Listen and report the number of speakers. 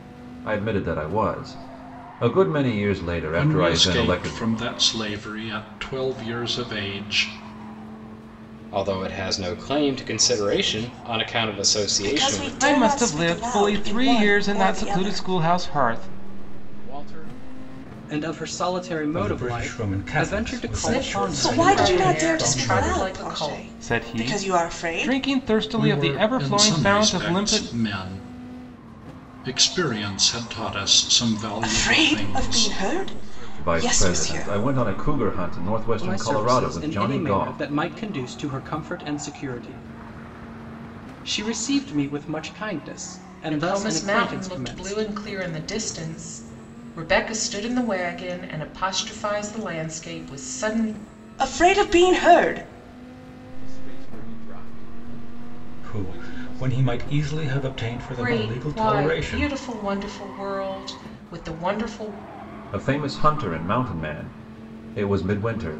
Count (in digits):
9